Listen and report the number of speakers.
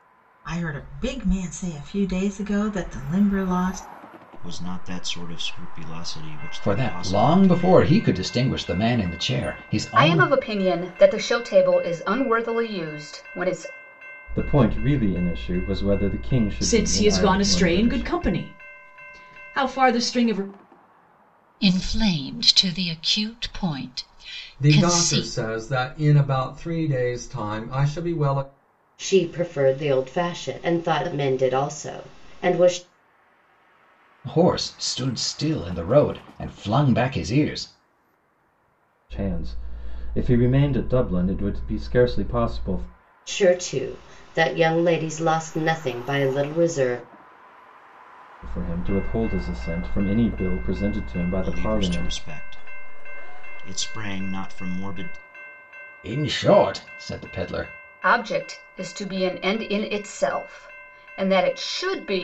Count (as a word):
nine